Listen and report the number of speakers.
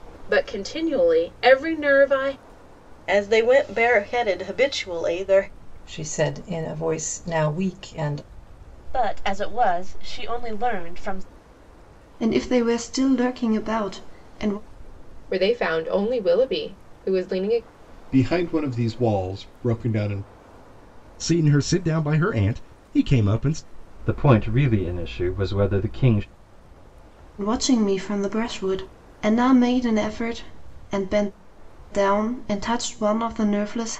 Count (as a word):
nine